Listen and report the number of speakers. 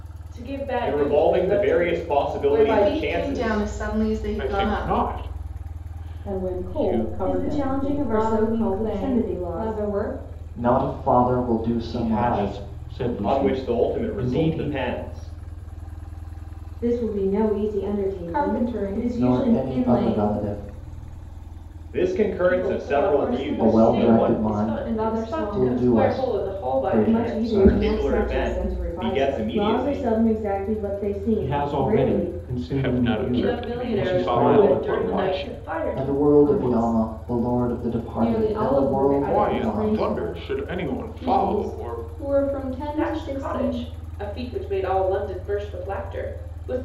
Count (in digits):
9